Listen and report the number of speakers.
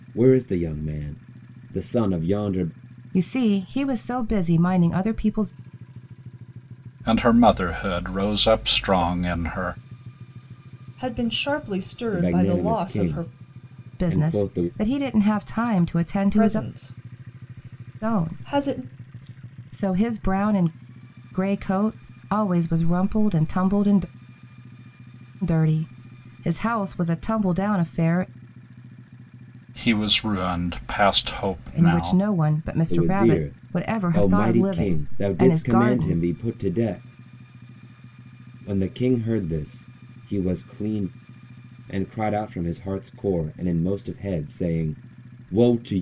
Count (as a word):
four